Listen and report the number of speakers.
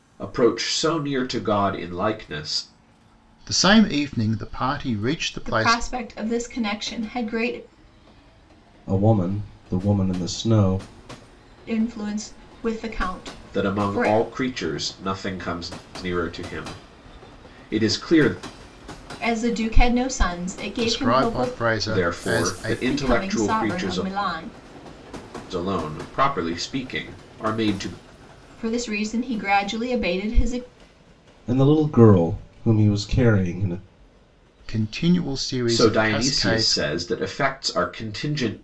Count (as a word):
four